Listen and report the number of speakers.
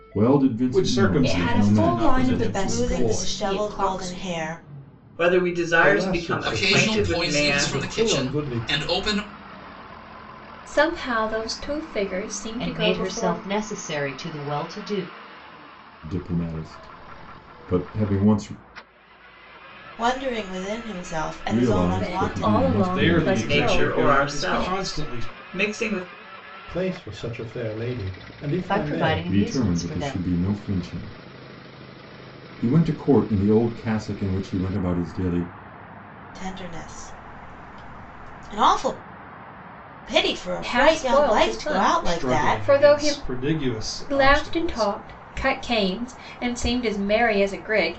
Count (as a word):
nine